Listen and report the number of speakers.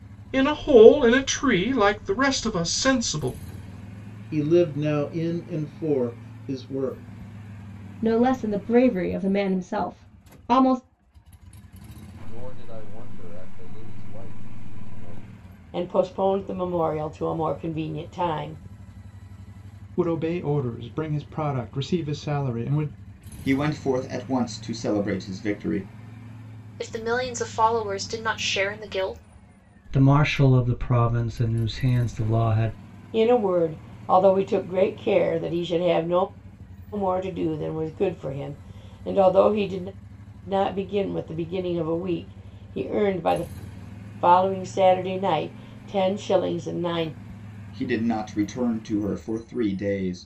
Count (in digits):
9